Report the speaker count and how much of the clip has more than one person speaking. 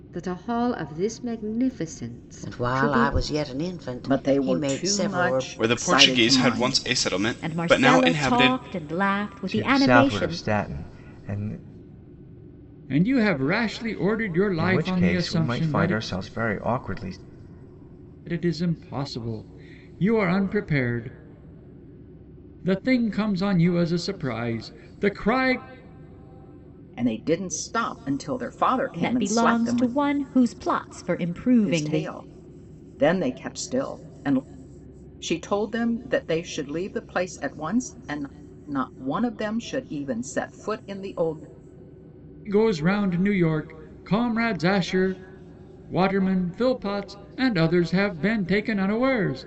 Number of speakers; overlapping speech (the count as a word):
seven, about 18%